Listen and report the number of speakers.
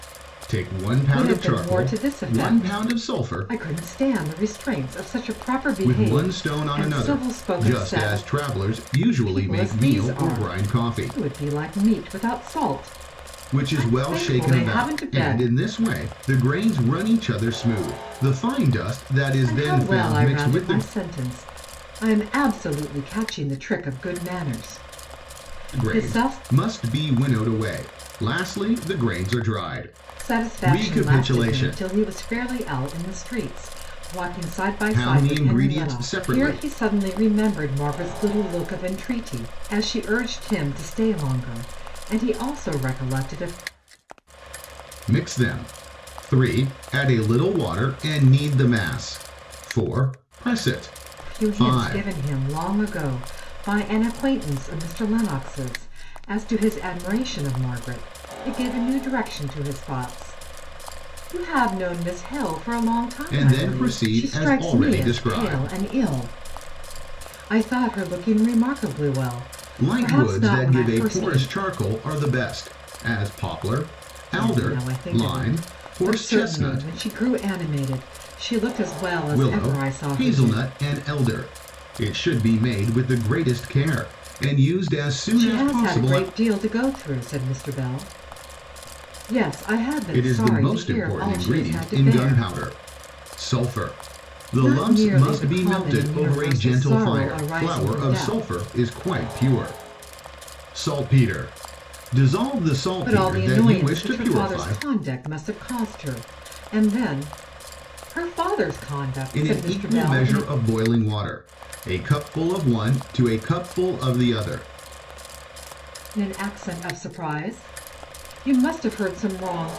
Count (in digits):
2